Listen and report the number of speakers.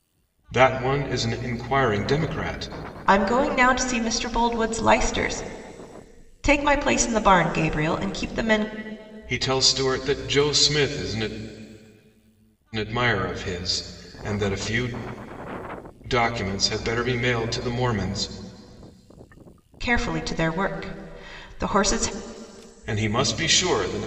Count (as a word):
two